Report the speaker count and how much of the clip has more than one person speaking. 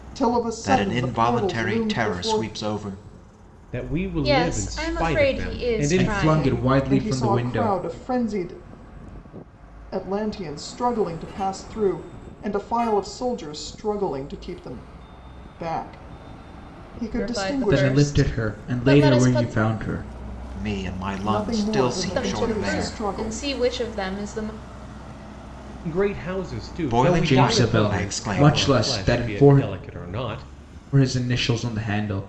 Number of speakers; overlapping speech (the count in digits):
5, about 40%